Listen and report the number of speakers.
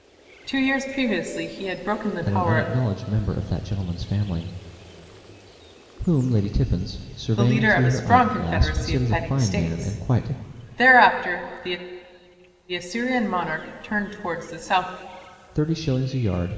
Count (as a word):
two